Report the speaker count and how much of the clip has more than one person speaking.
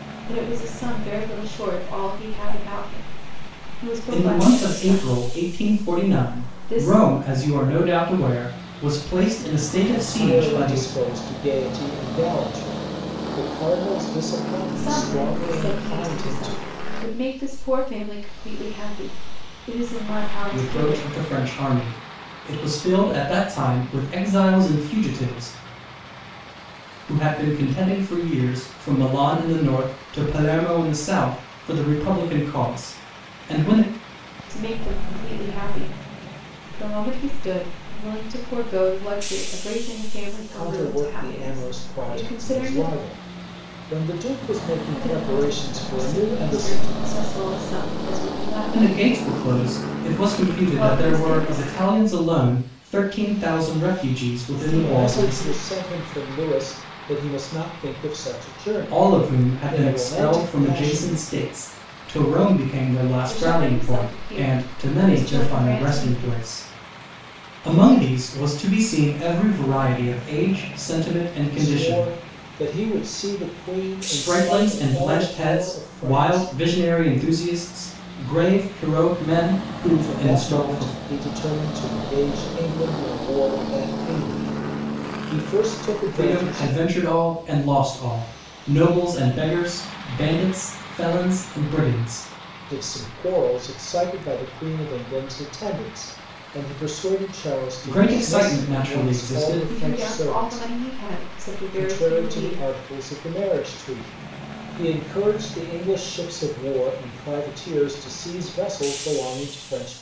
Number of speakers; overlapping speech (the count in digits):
3, about 26%